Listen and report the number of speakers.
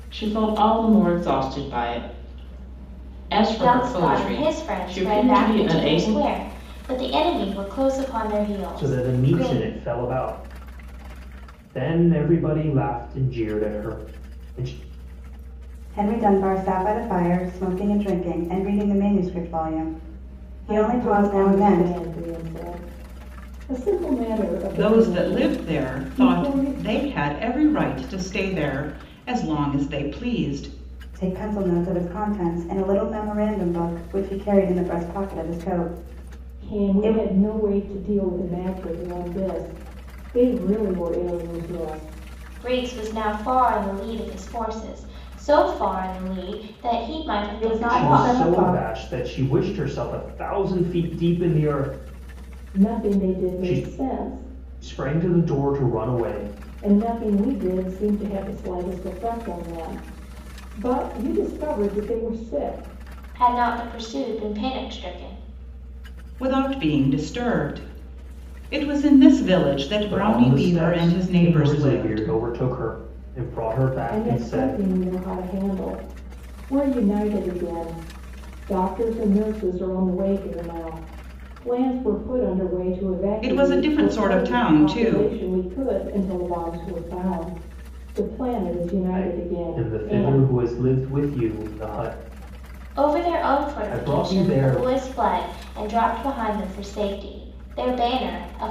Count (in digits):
6